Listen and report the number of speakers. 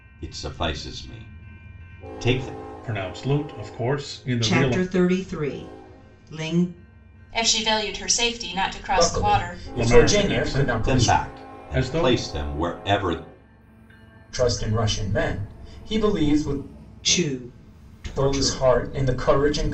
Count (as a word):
five